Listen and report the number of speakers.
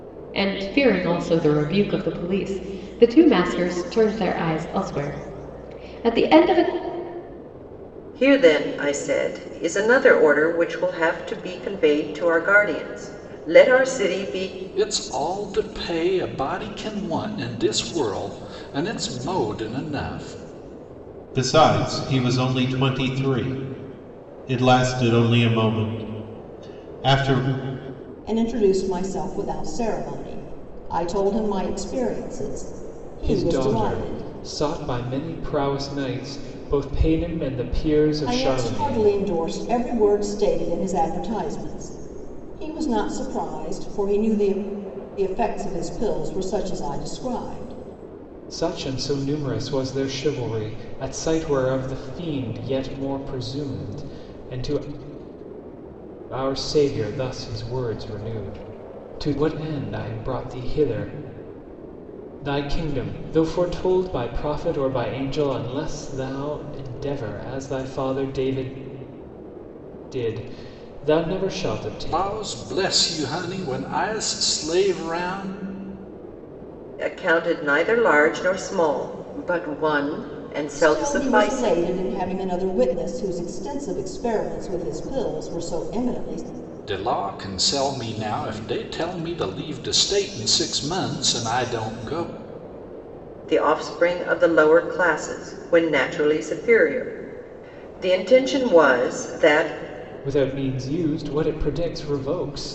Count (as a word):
six